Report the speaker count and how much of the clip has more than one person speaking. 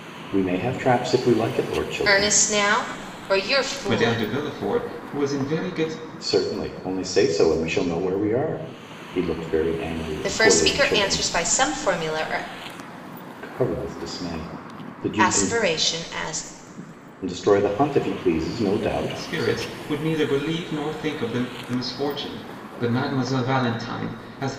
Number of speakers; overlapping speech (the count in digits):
3, about 12%